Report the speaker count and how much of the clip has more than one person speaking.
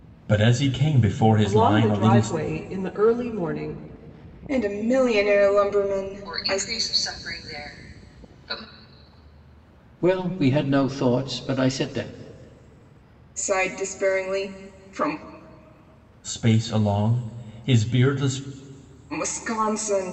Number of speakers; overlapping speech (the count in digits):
5, about 7%